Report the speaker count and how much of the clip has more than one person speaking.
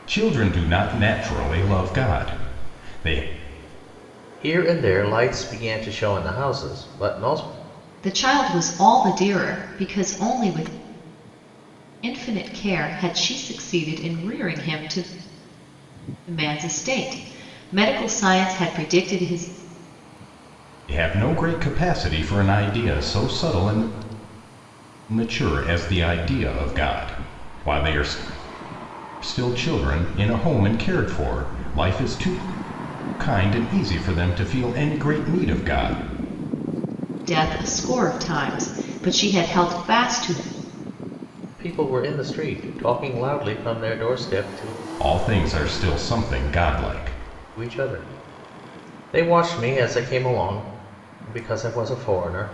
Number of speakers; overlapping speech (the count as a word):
three, no overlap